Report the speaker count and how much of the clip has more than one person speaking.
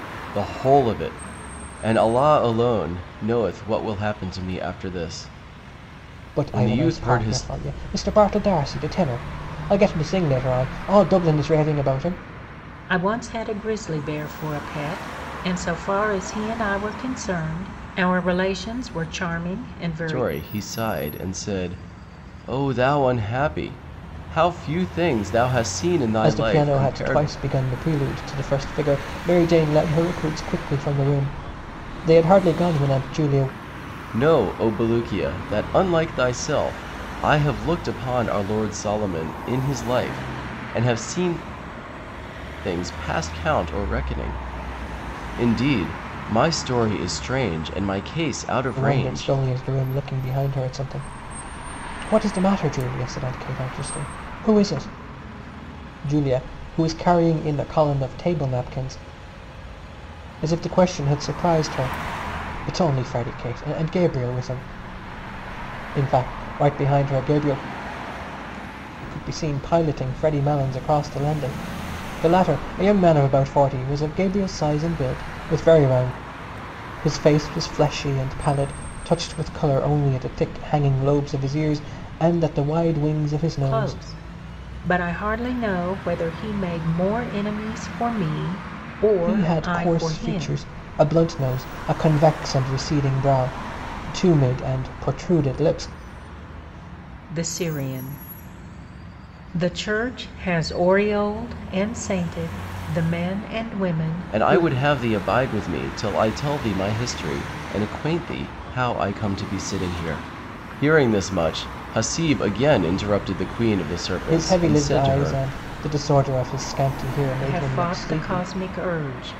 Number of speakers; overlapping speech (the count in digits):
3, about 7%